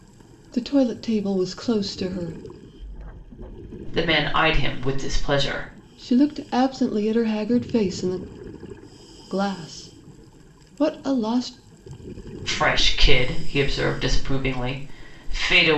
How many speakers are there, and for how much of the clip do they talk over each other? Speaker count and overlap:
2, no overlap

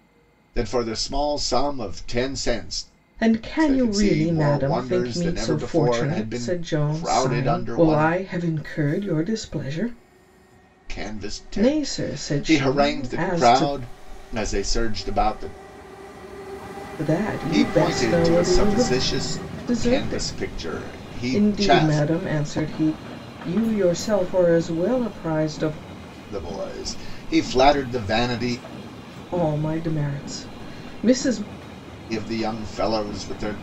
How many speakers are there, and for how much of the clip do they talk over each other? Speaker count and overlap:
2, about 29%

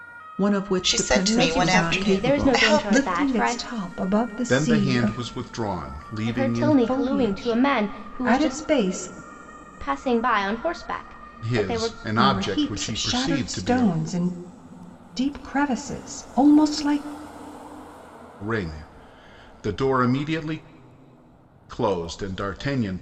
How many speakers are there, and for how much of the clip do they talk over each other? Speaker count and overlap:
5, about 37%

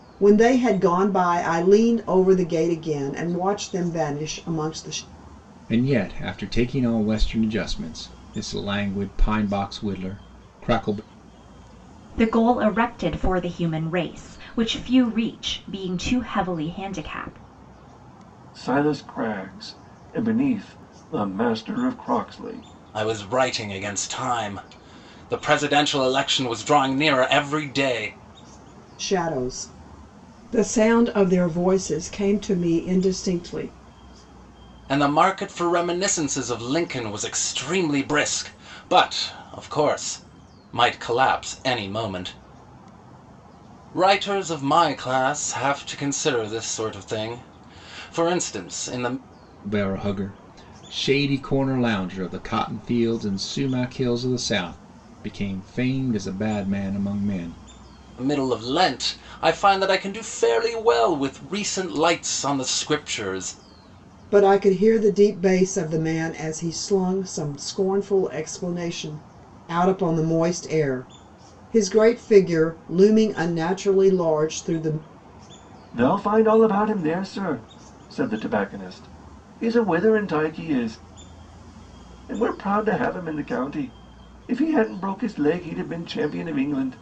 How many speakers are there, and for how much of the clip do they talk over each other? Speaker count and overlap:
5, no overlap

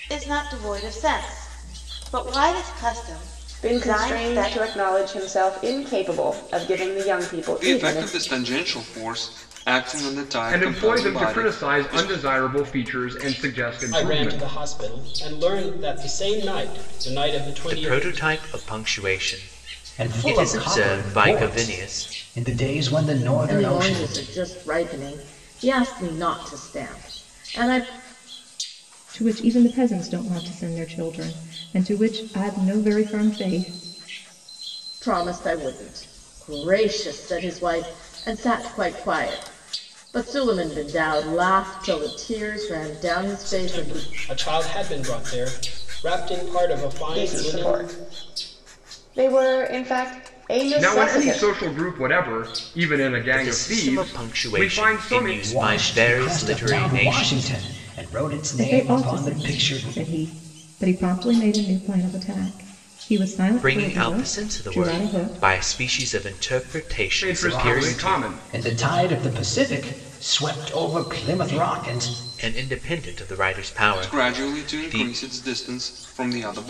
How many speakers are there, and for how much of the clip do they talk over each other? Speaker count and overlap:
9, about 25%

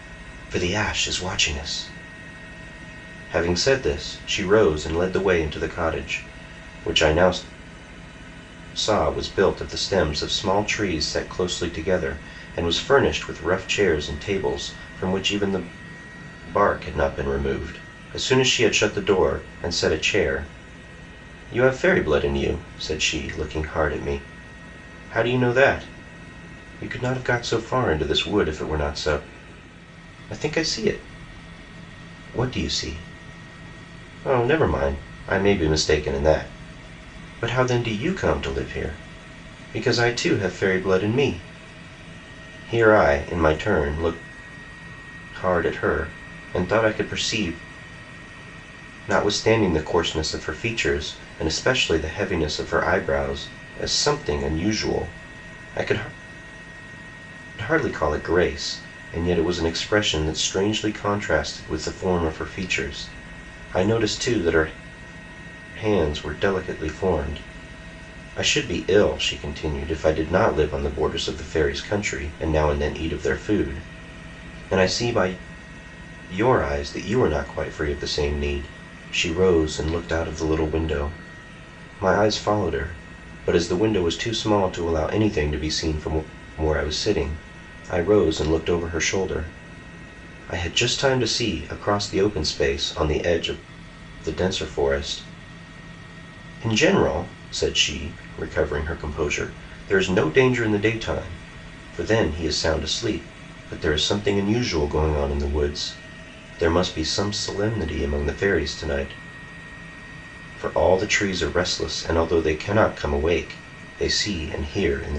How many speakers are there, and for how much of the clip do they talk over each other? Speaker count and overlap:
1, no overlap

